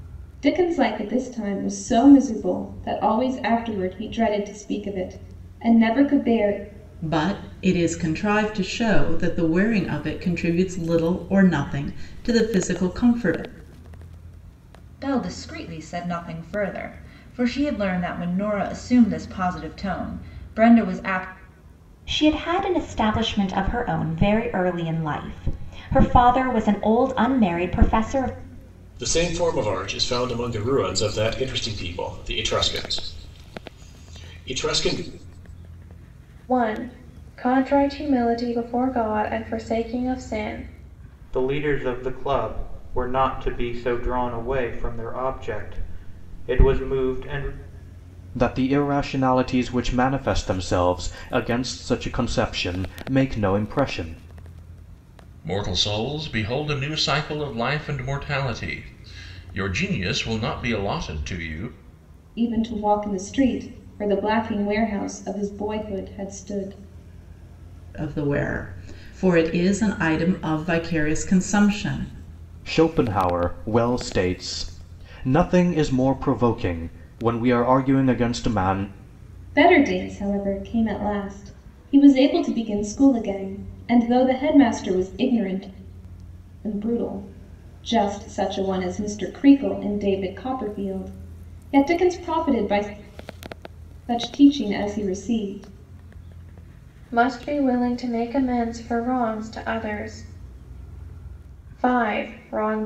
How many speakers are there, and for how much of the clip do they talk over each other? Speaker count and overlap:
9, no overlap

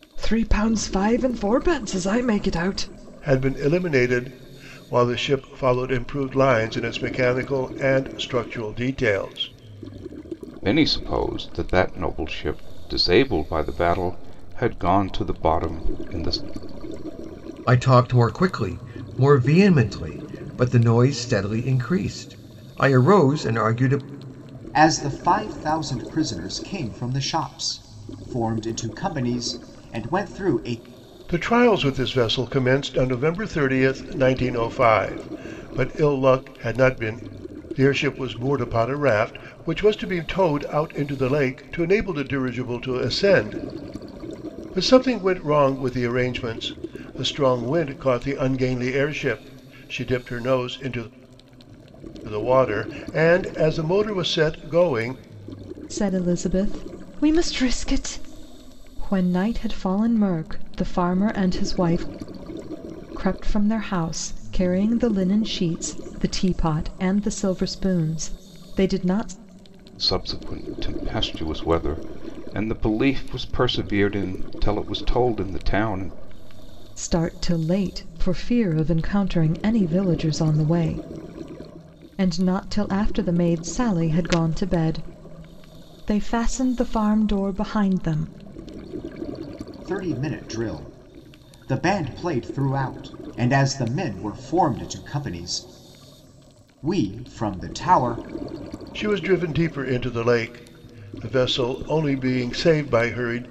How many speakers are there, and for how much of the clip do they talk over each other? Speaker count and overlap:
5, no overlap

